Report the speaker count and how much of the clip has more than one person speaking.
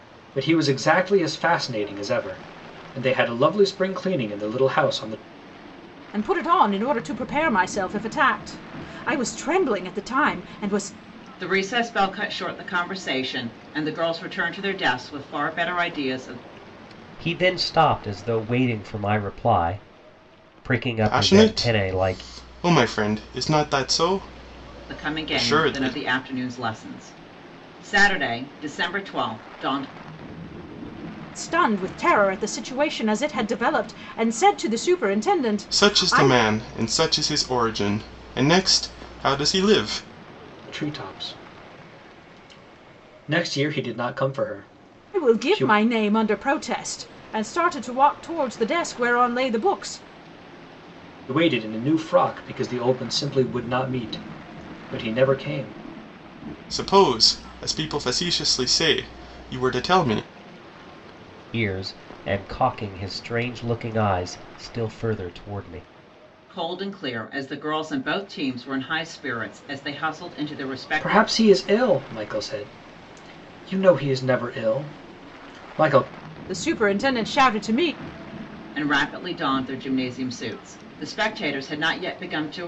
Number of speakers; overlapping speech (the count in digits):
5, about 5%